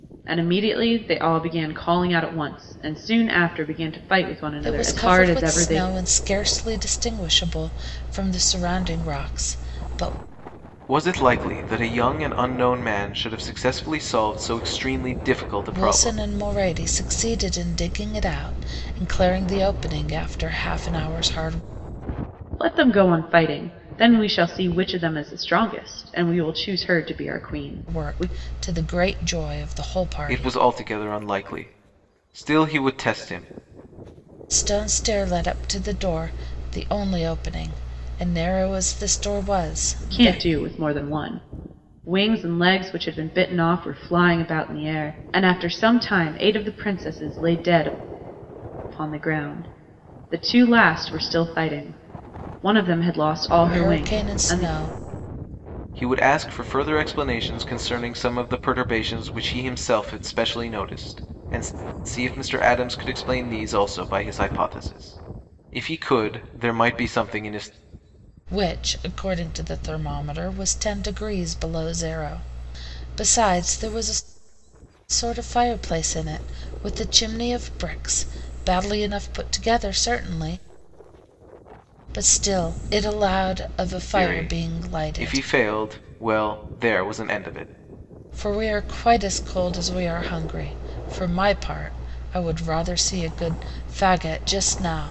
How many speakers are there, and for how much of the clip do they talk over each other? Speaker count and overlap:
3, about 6%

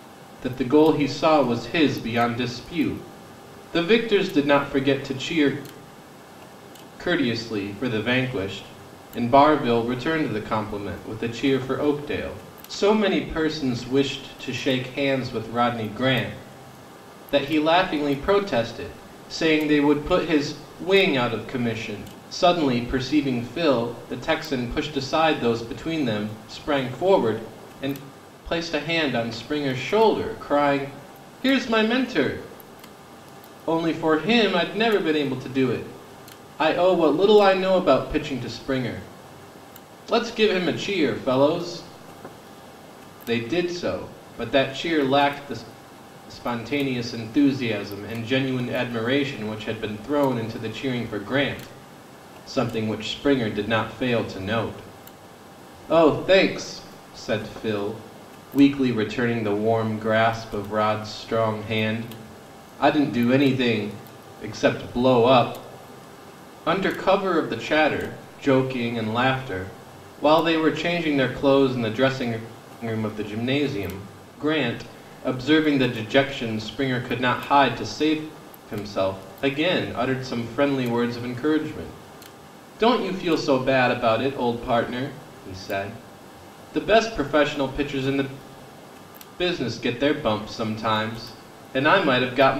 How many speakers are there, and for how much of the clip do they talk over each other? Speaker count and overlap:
1, no overlap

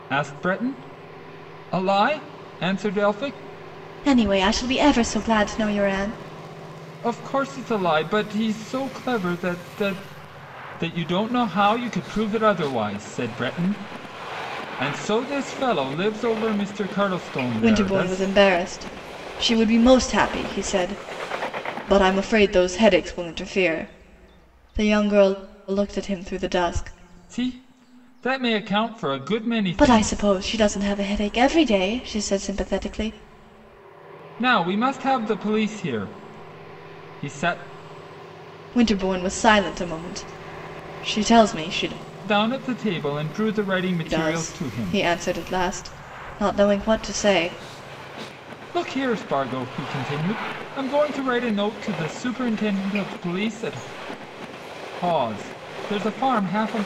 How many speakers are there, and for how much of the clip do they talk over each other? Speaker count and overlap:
2, about 4%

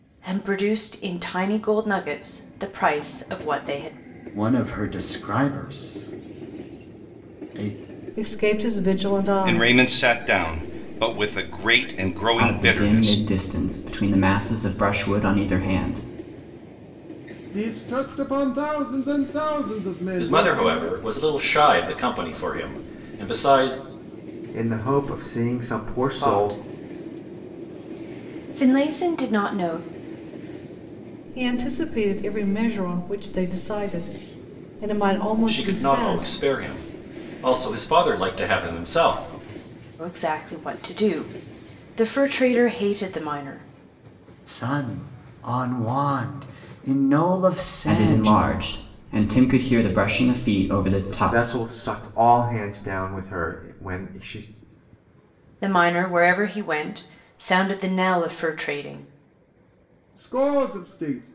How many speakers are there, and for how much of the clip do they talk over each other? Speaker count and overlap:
8, about 7%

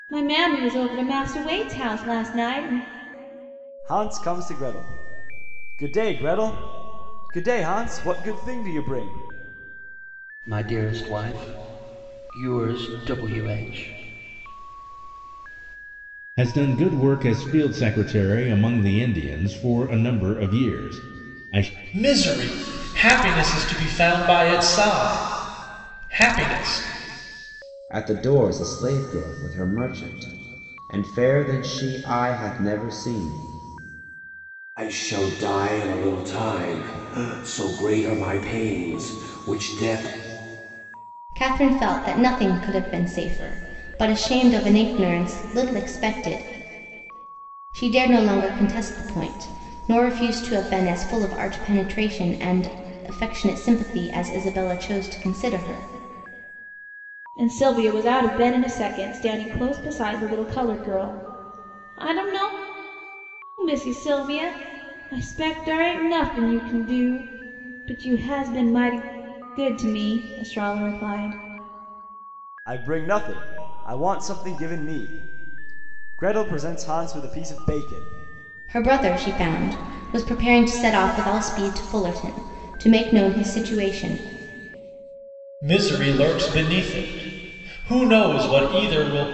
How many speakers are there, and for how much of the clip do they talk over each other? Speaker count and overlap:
8, no overlap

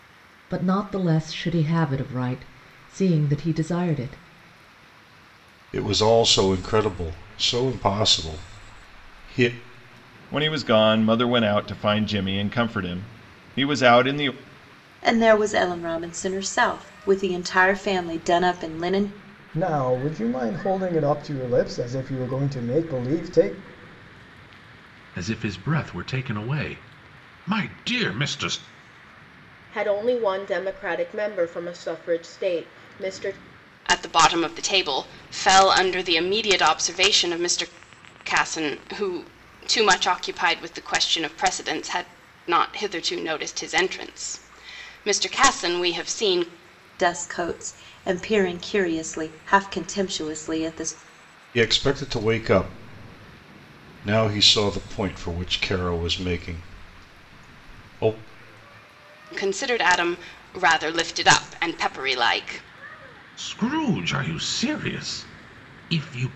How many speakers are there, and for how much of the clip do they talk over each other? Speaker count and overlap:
8, no overlap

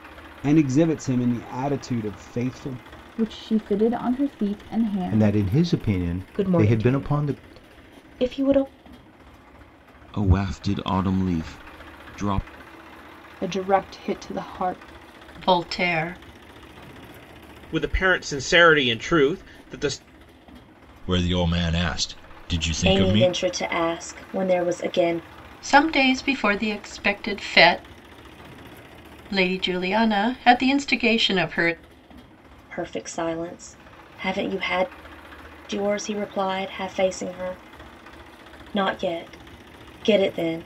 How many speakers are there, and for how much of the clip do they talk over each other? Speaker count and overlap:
10, about 5%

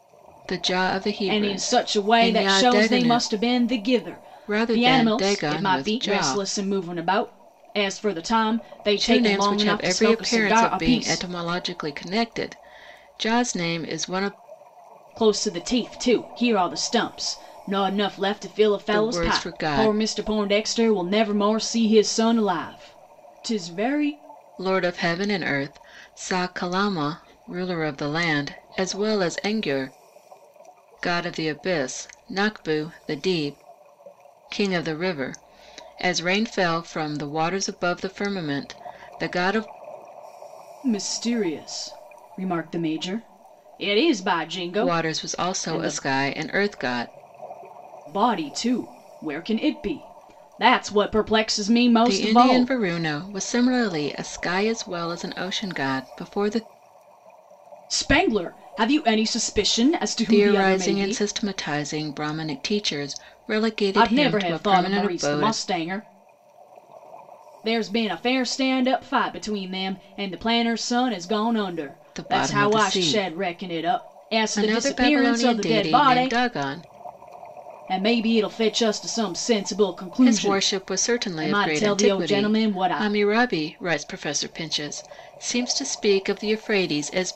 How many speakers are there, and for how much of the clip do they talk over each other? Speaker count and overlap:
2, about 20%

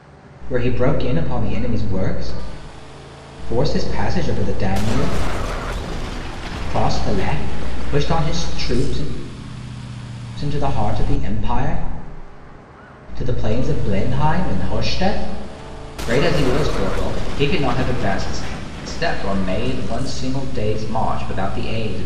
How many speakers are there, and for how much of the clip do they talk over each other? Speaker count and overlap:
1, no overlap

